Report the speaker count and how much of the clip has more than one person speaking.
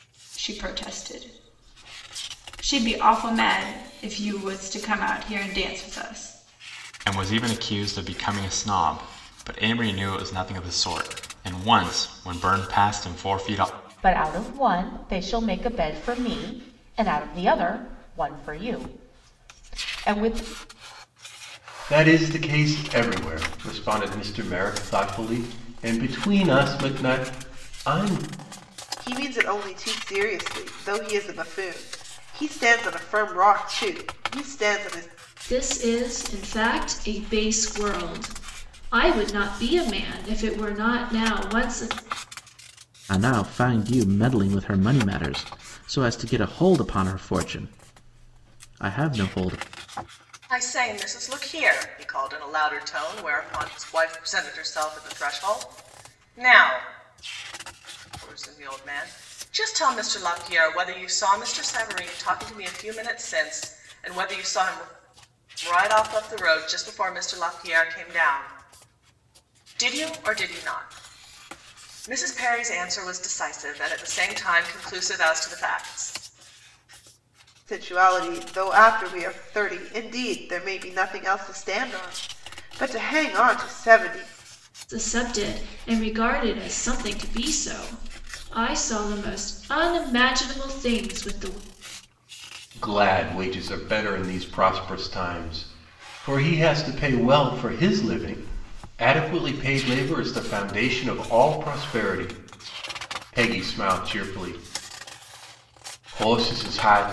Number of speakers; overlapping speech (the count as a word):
eight, no overlap